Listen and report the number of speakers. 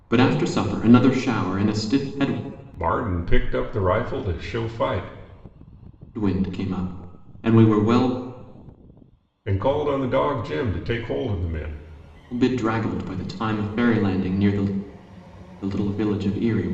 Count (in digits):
2